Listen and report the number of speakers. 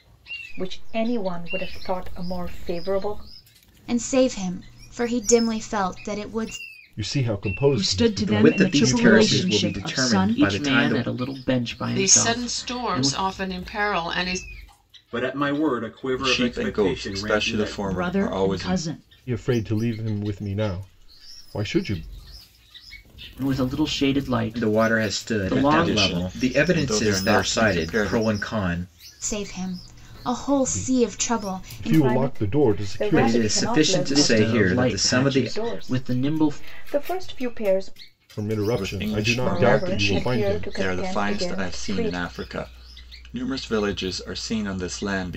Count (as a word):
nine